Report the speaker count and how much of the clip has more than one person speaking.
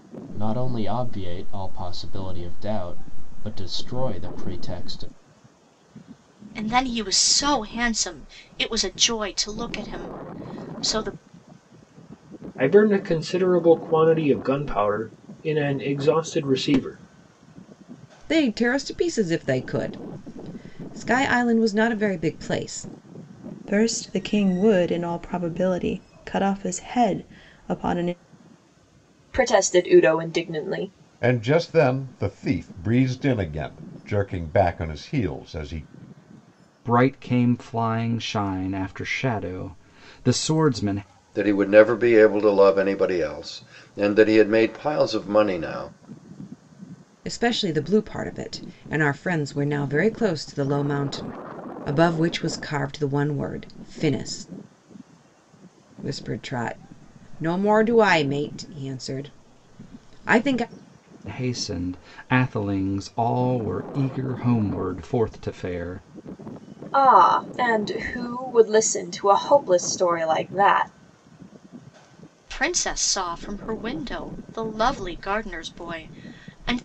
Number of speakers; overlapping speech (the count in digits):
9, no overlap